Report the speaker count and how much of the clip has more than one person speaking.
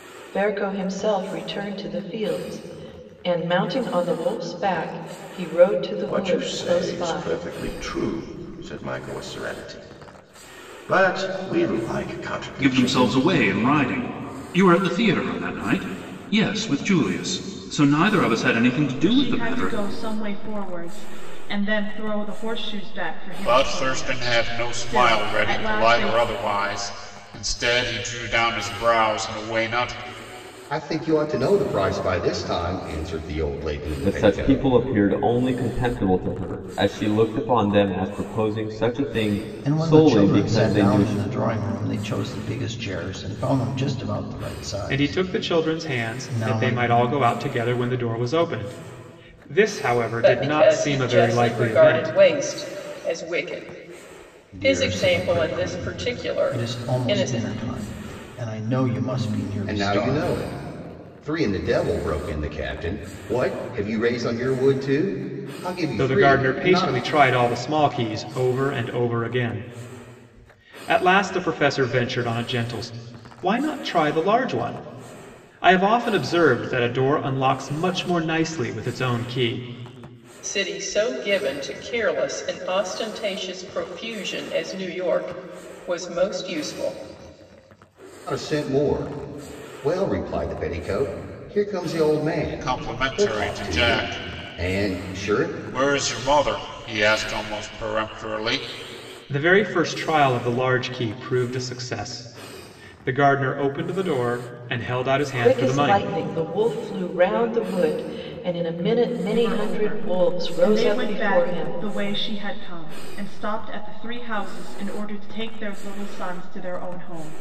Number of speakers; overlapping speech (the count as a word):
ten, about 20%